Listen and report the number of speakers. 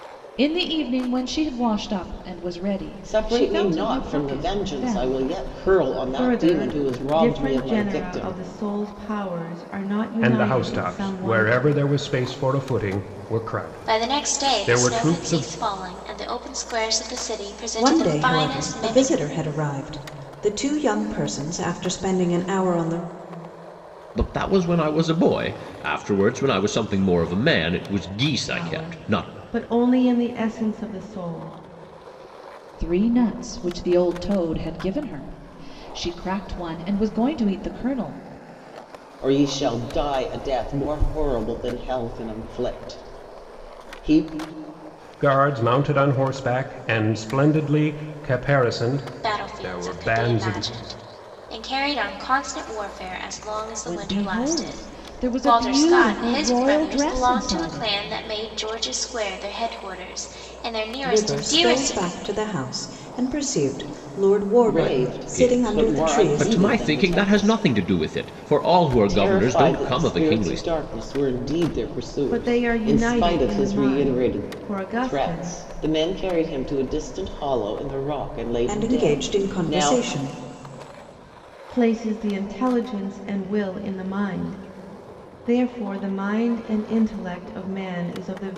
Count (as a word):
seven